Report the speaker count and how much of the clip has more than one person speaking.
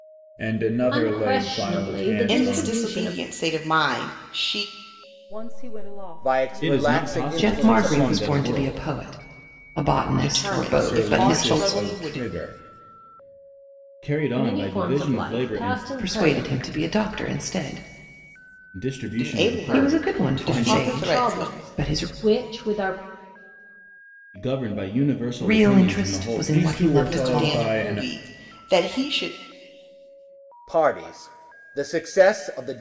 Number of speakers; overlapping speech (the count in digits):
7, about 45%